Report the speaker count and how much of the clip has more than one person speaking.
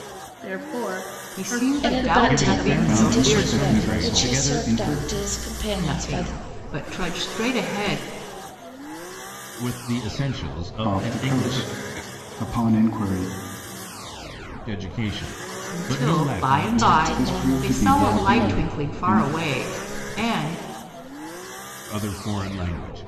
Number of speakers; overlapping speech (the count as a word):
five, about 38%